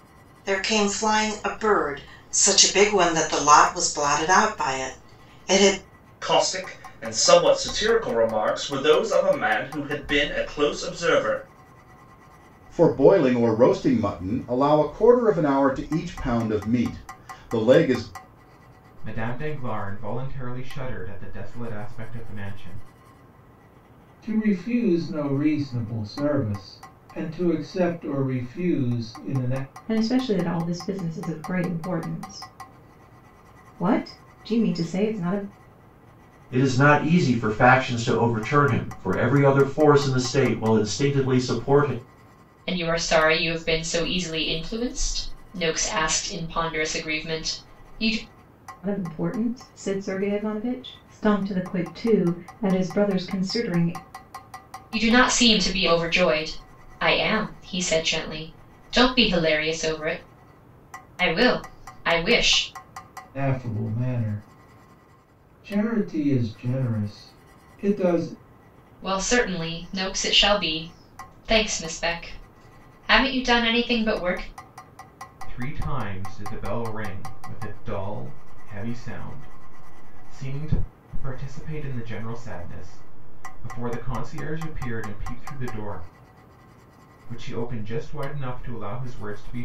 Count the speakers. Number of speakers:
8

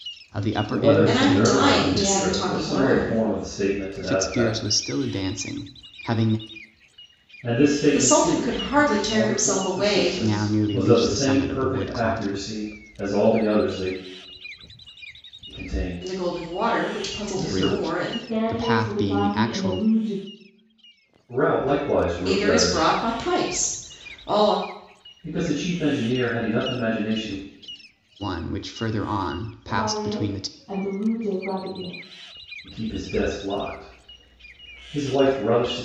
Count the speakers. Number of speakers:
4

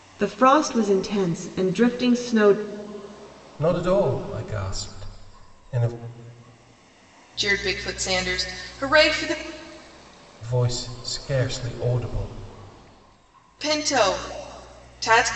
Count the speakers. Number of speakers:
3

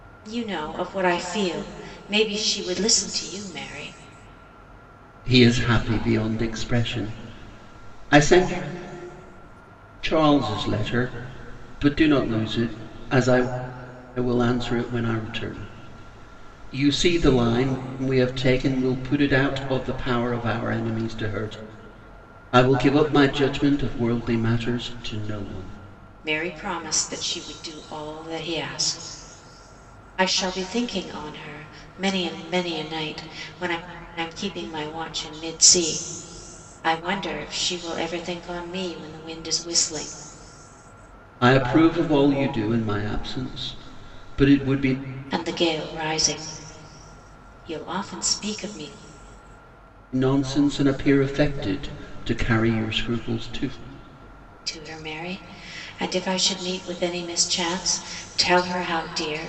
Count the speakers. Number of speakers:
2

